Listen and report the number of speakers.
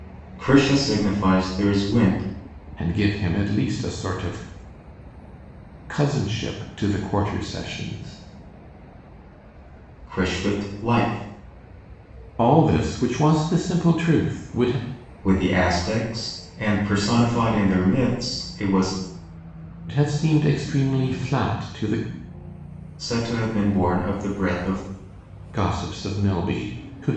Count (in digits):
2